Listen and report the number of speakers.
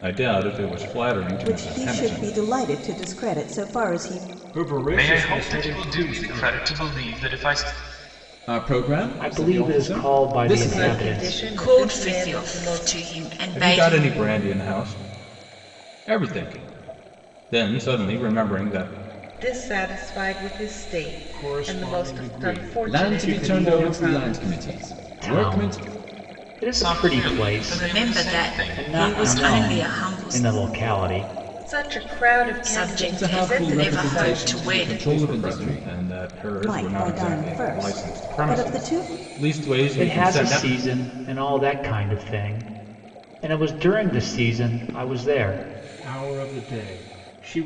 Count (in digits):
8